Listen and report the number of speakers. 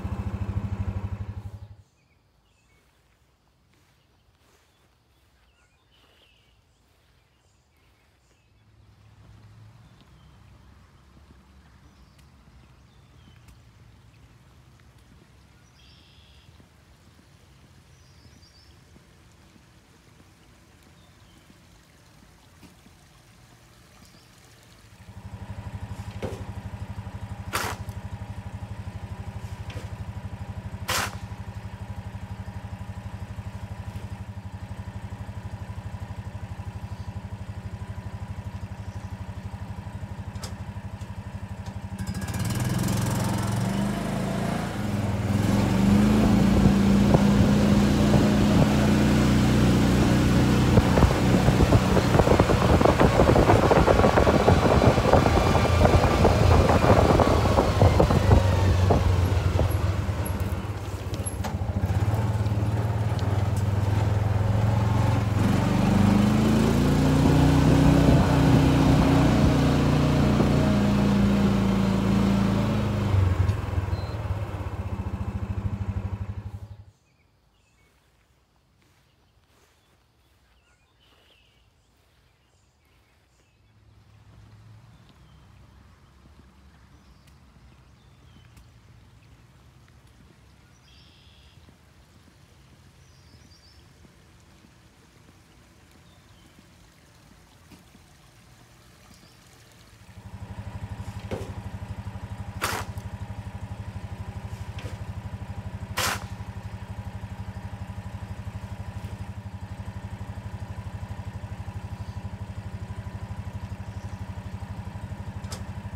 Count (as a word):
zero